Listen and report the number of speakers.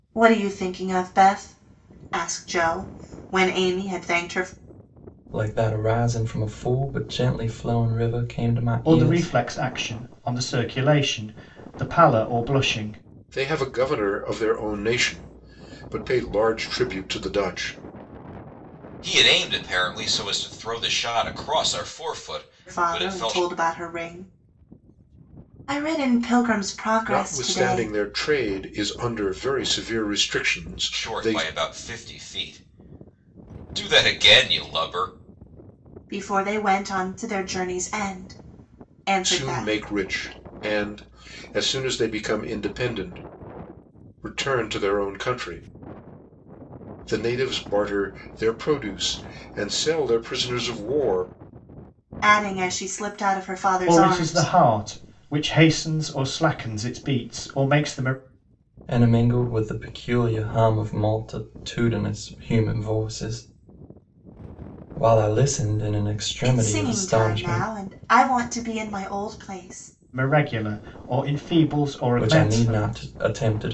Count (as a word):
five